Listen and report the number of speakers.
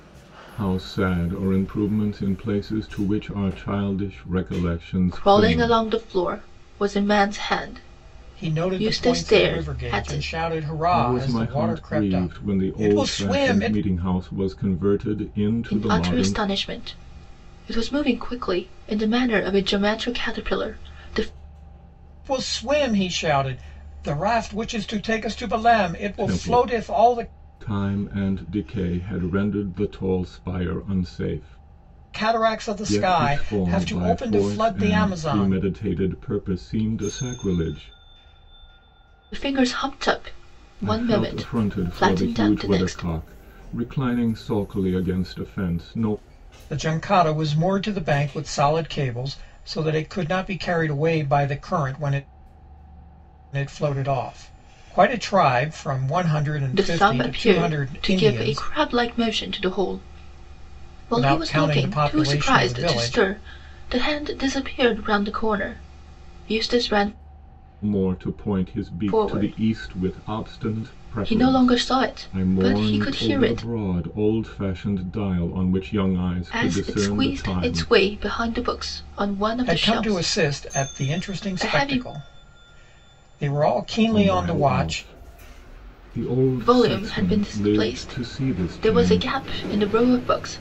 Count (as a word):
three